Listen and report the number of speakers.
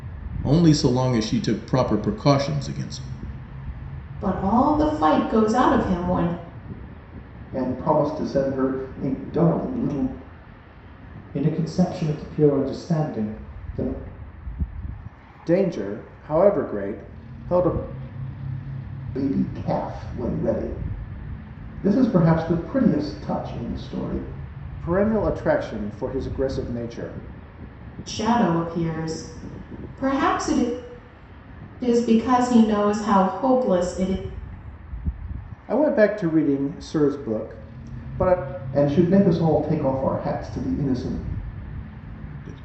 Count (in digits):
5